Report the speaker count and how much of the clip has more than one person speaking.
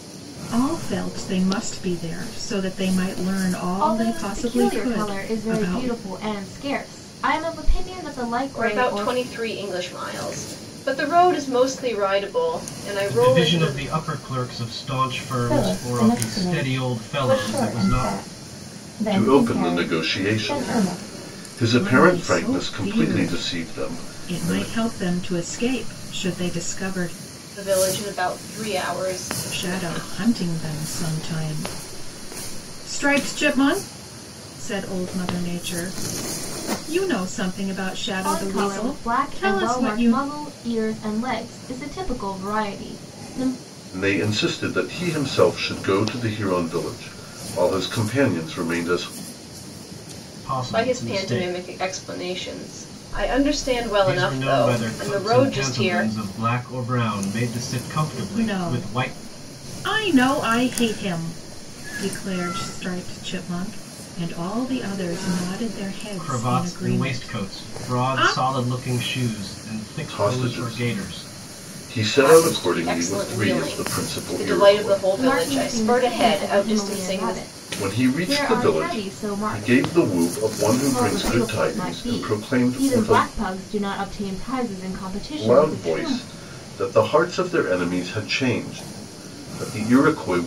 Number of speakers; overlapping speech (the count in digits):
6, about 35%